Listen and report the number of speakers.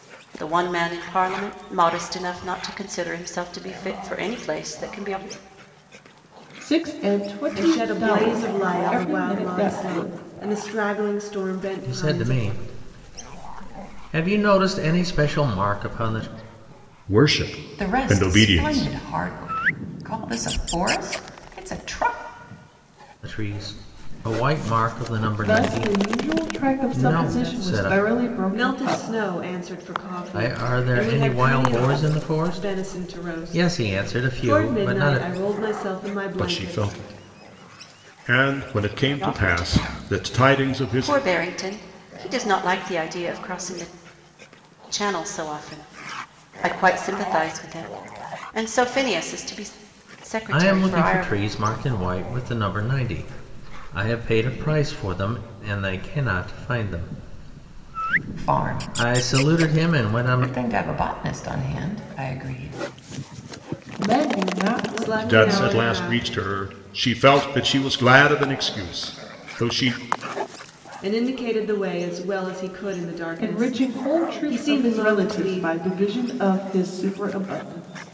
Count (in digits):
6